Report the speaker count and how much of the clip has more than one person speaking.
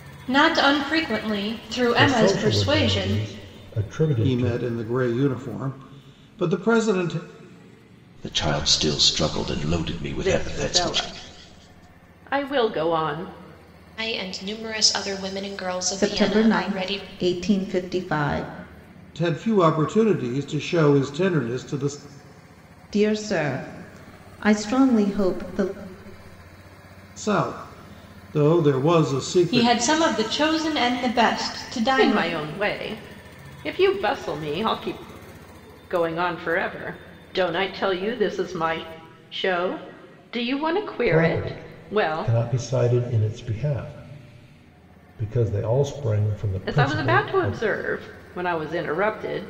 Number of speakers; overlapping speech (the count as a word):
seven, about 14%